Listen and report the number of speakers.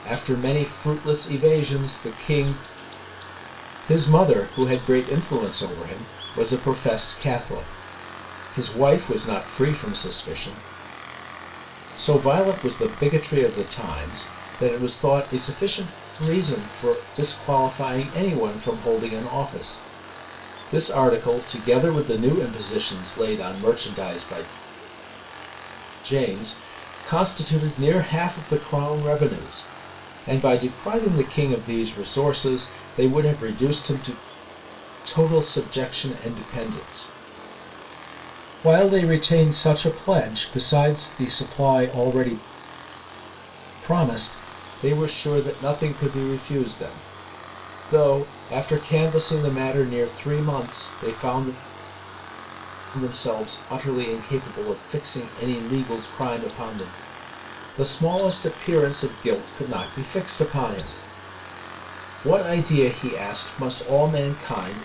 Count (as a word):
one